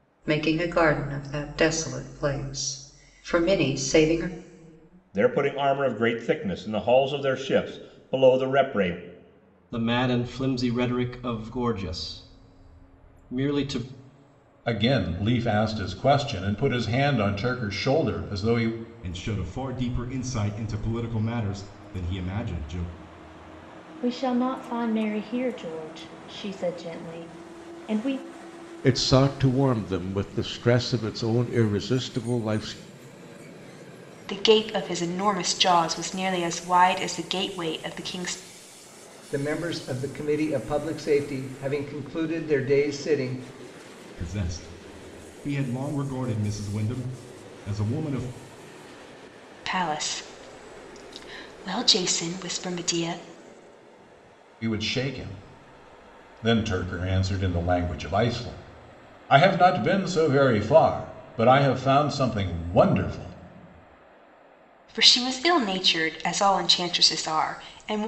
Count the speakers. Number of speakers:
nine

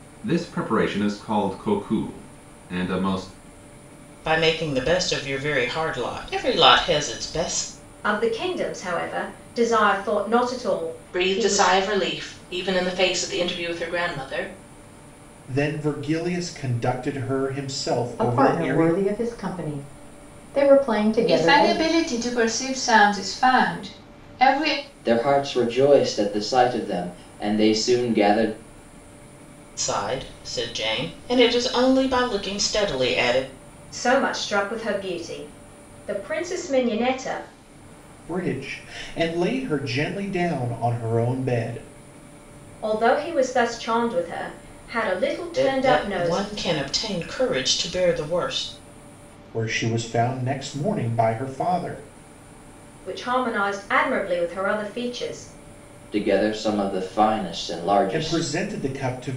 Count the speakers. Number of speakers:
eight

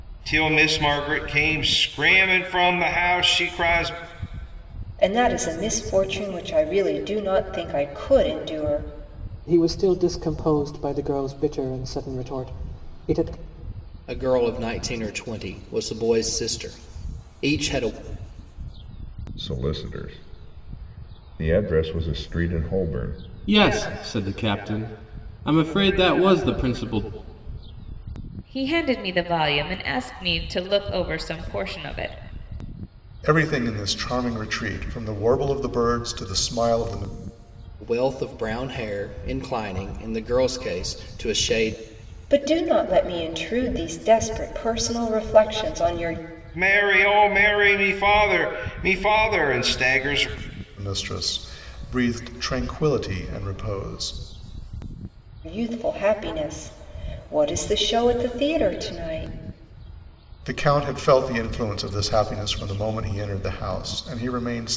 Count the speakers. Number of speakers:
eight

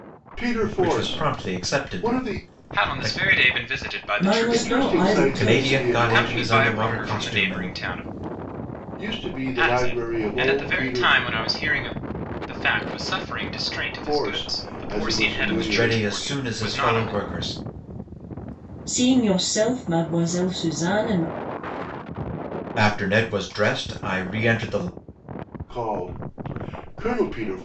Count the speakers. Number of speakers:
four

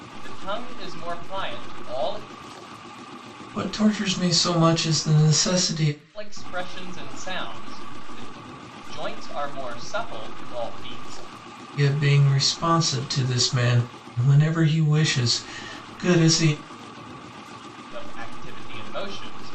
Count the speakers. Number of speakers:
two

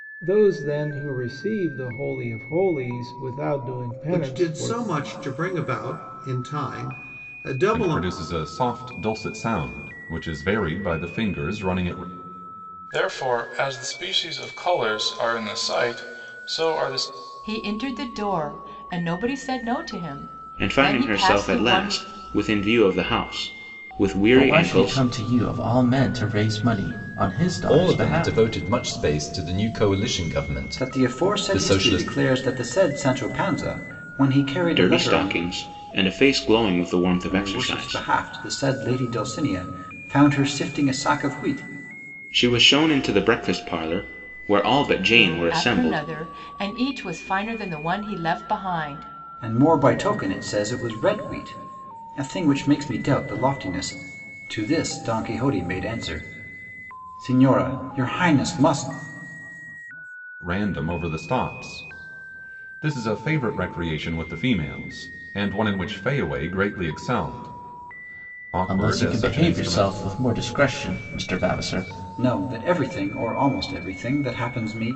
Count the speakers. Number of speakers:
nine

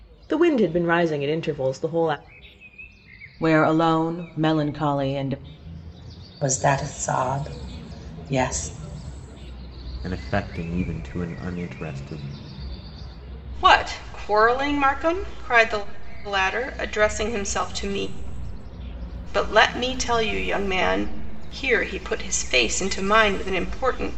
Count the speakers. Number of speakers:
five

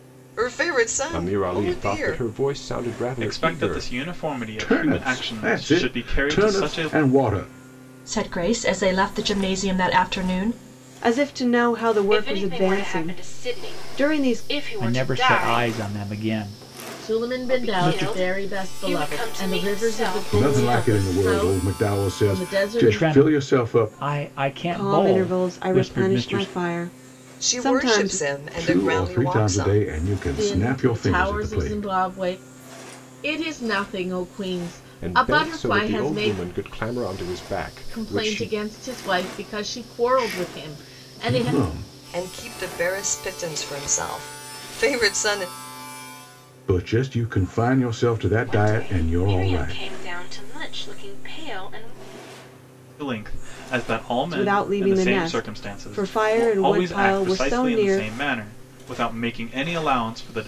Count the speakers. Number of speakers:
nine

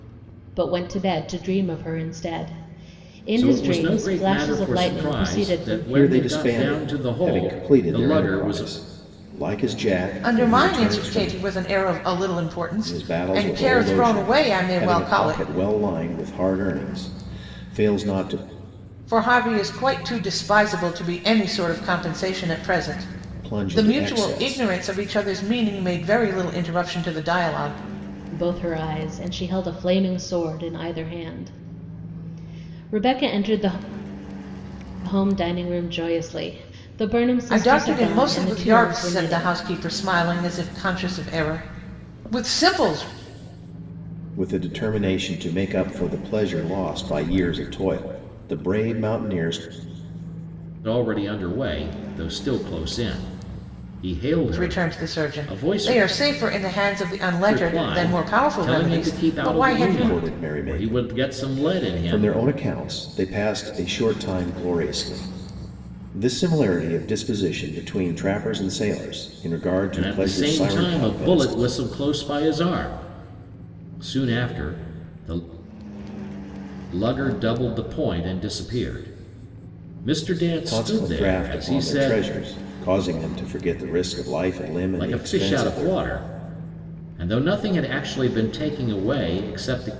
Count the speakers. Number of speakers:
four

